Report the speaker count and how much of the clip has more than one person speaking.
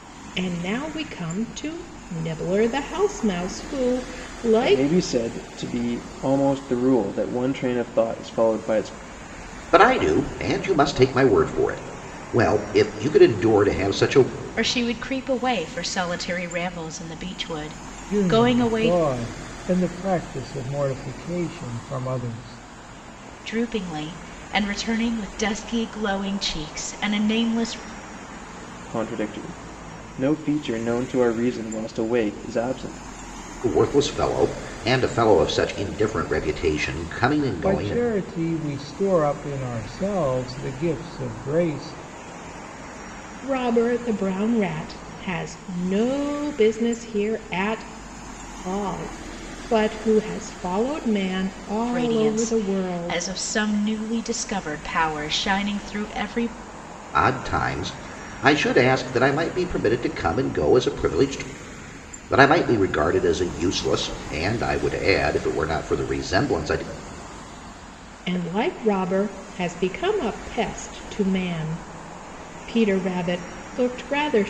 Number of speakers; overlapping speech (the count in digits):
5, about 4%